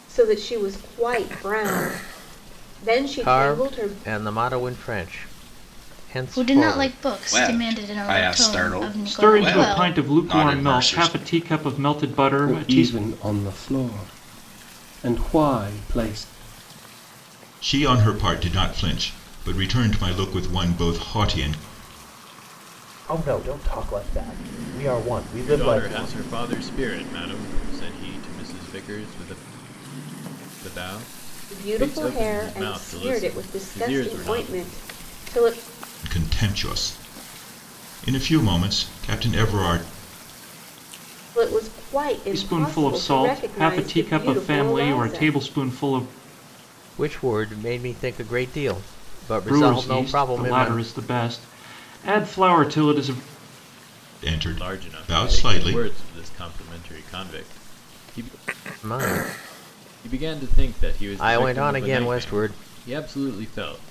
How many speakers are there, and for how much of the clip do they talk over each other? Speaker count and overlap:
9, about 28%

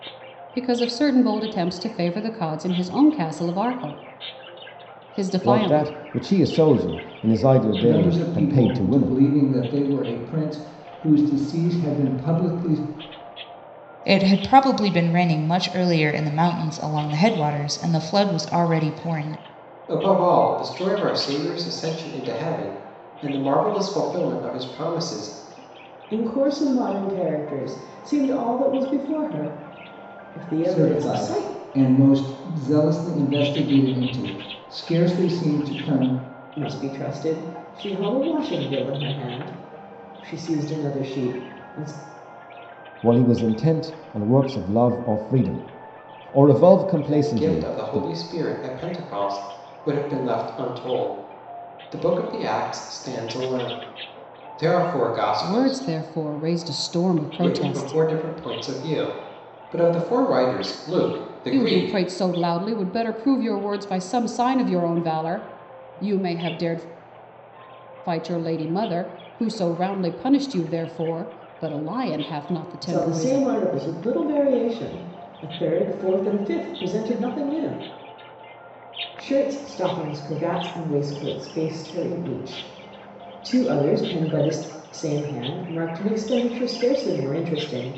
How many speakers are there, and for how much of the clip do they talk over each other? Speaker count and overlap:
6, about 7%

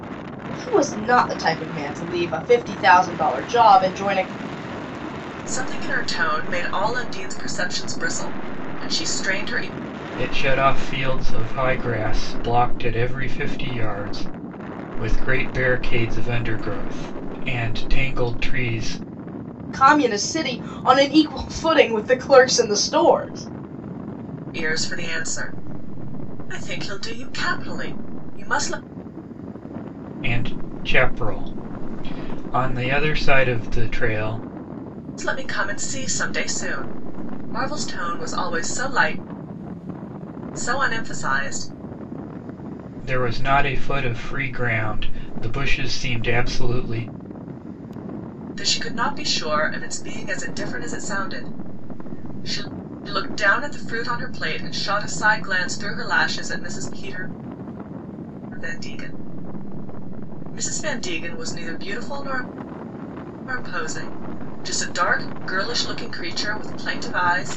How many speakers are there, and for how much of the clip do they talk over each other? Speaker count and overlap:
3, no overlap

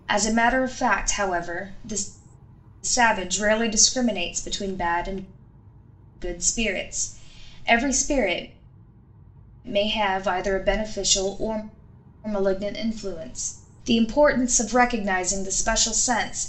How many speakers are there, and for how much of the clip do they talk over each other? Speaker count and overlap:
1, no overlap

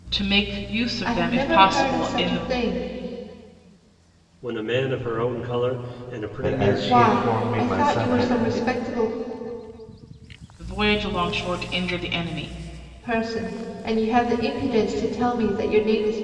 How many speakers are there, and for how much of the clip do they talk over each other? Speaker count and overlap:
4, about 23%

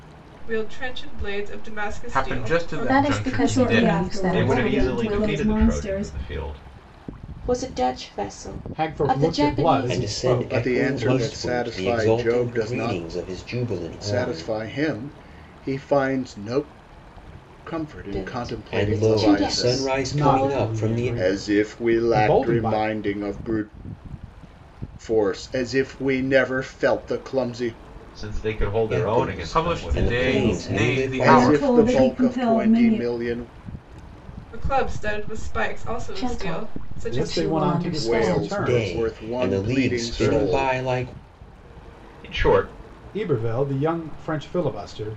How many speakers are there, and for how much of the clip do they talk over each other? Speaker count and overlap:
9, about 51%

